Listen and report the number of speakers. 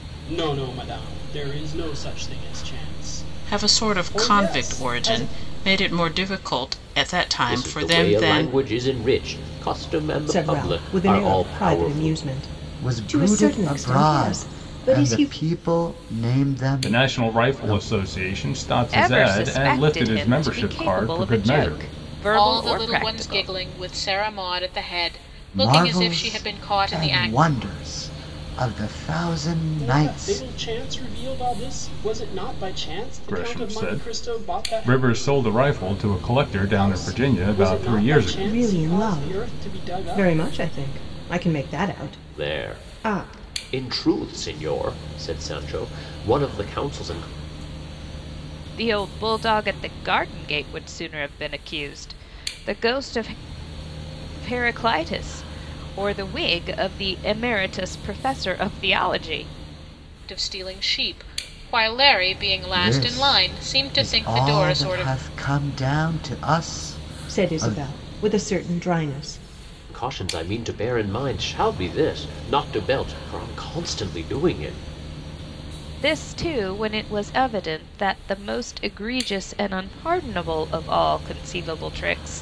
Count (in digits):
8